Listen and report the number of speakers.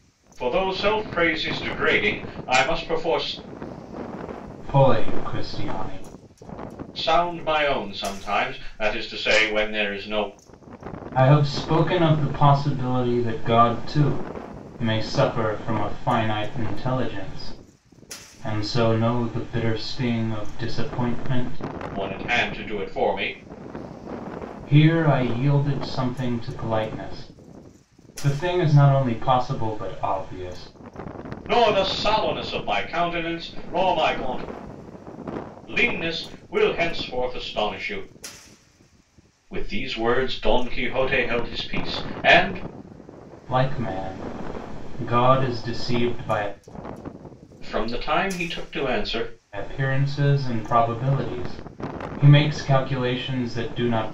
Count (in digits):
2